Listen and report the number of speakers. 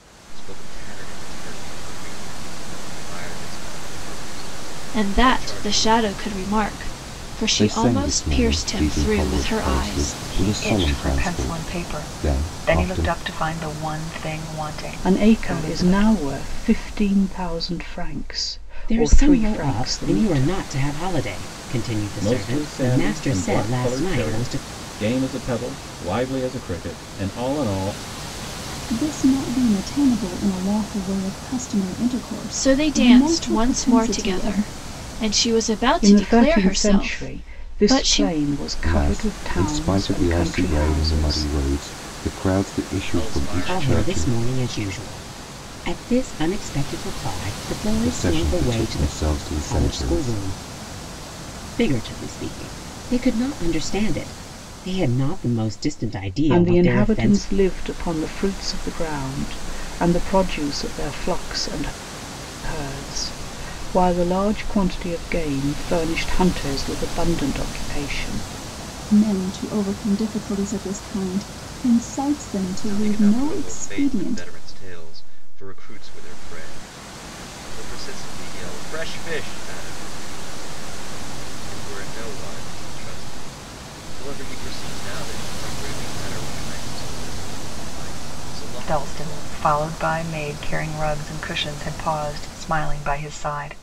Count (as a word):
eight